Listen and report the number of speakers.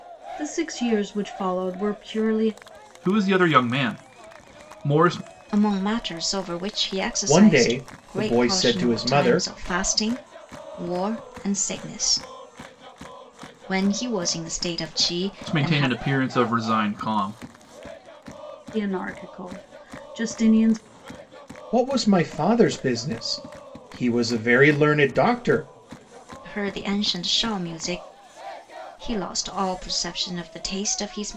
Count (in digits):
4